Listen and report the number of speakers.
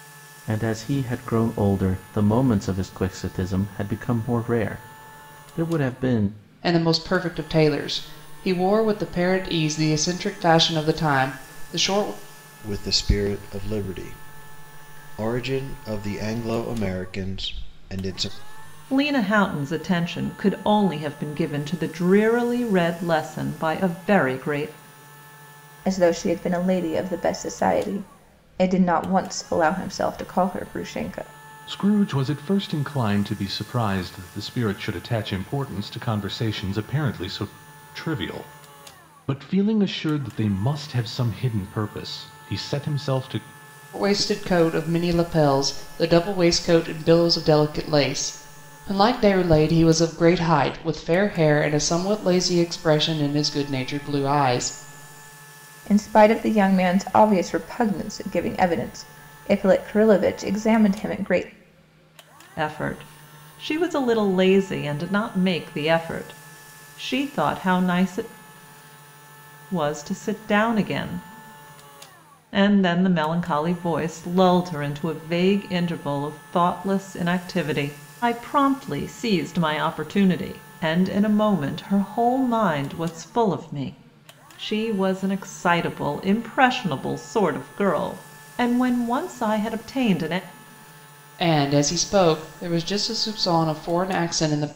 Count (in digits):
6